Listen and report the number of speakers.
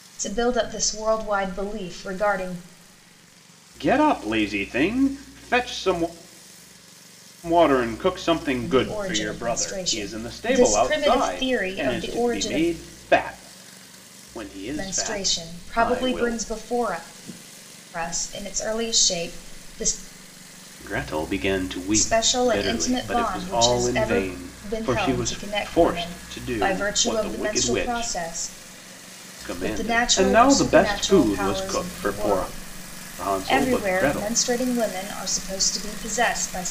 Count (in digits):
2